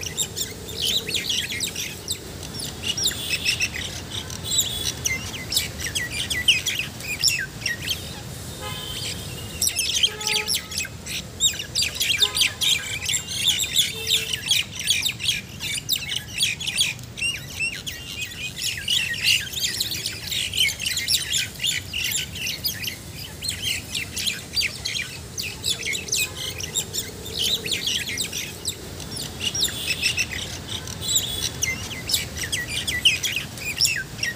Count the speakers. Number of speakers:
zero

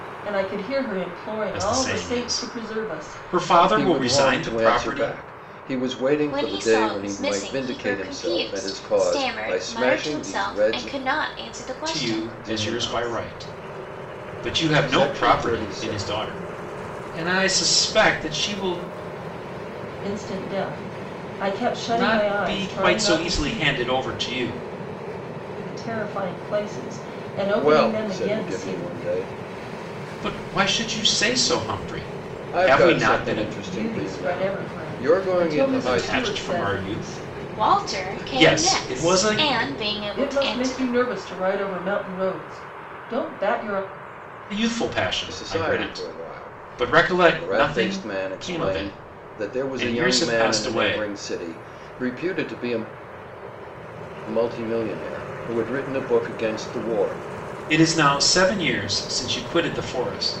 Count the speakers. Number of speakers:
four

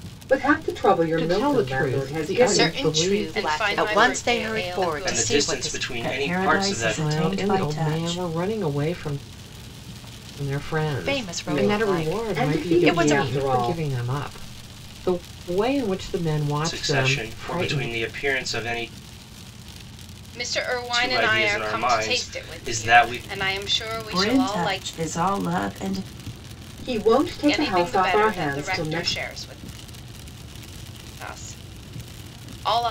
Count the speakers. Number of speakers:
seven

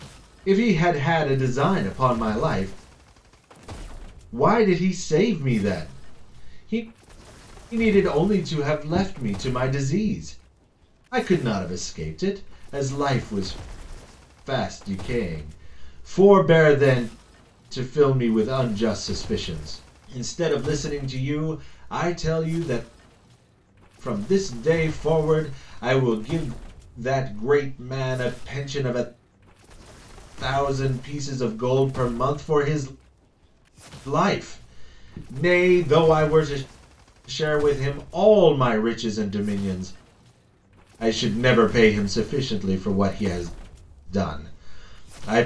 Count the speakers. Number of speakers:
one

